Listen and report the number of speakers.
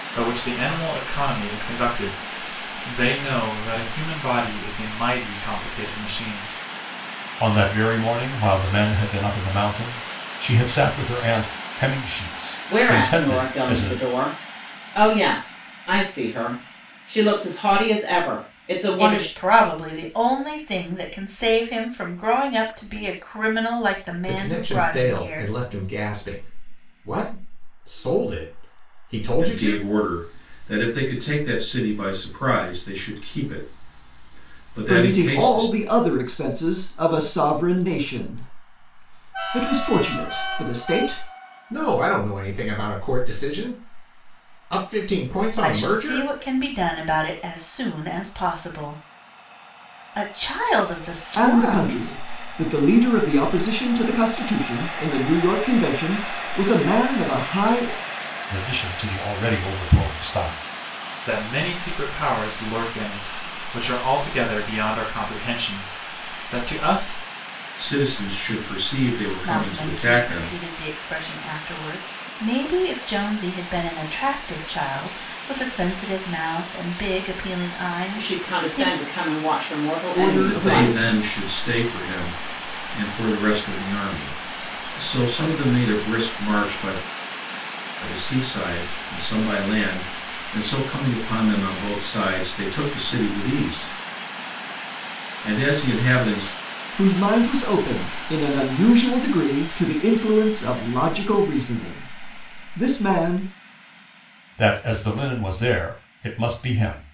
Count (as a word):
seven